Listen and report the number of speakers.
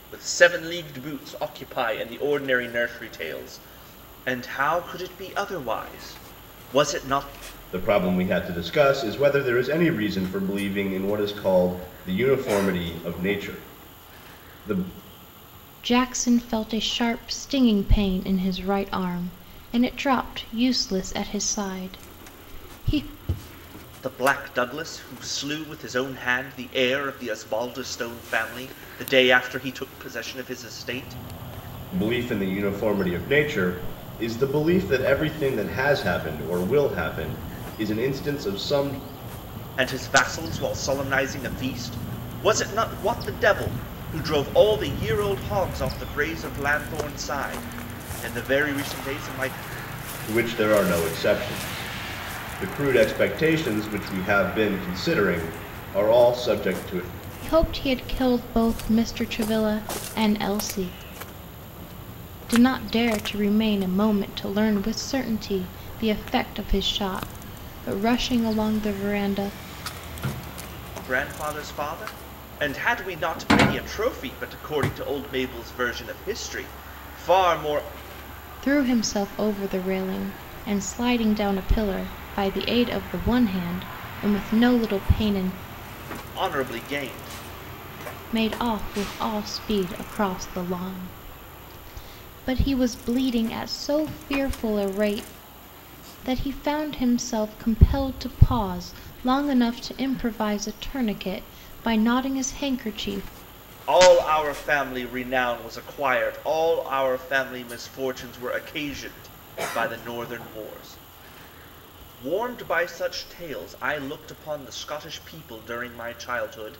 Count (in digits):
3